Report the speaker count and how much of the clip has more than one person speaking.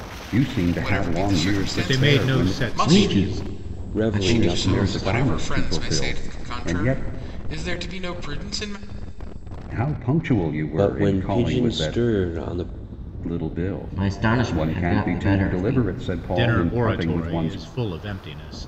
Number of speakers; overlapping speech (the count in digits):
5, about 56%